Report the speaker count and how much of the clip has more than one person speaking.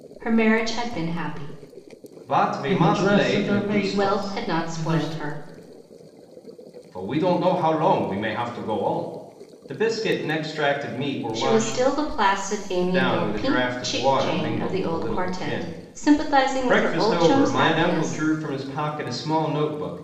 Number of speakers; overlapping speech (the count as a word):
three, about 40%